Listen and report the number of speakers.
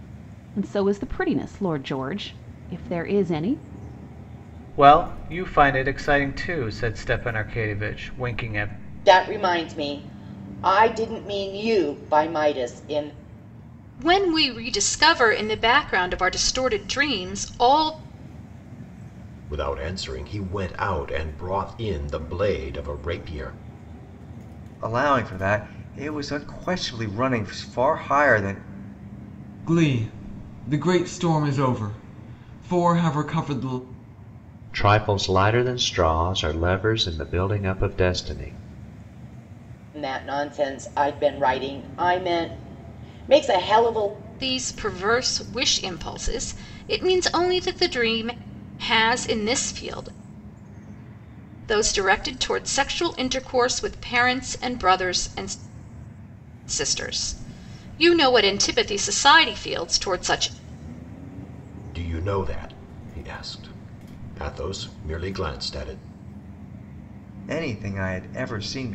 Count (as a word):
eight